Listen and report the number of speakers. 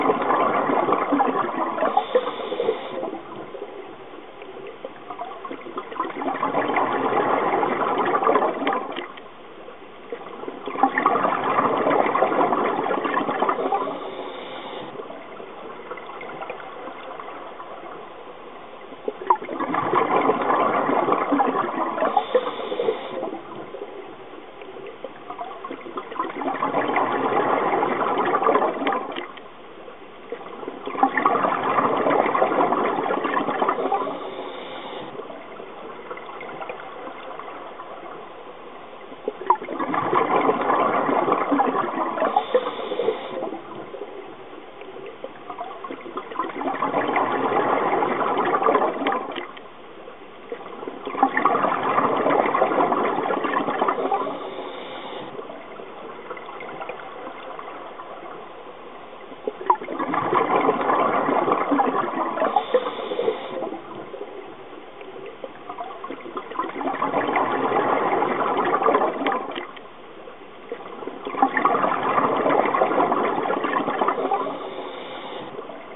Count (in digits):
0